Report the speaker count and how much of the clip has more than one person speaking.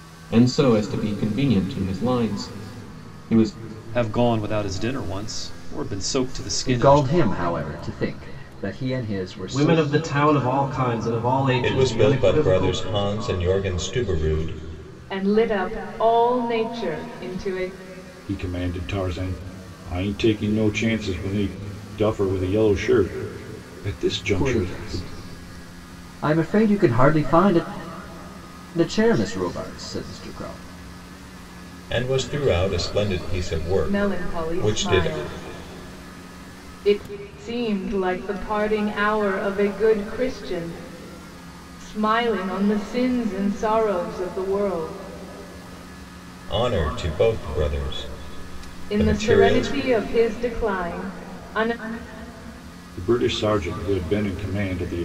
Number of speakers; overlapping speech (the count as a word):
seven, about 9%